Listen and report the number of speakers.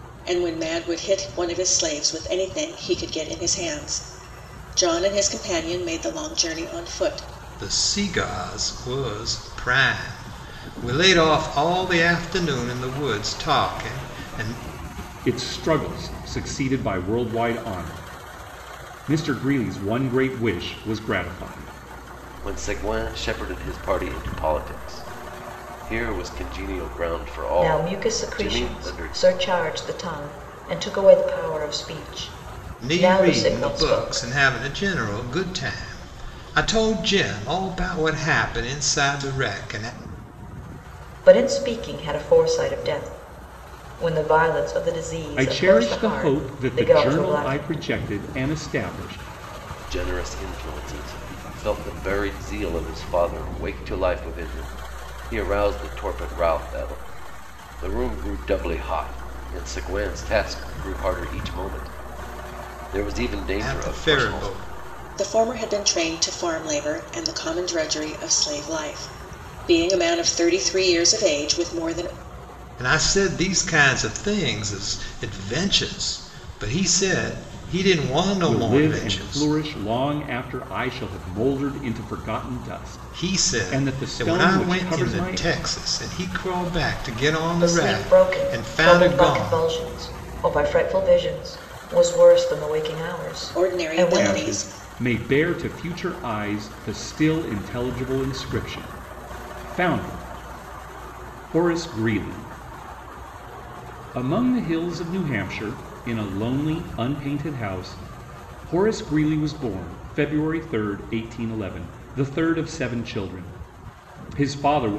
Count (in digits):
5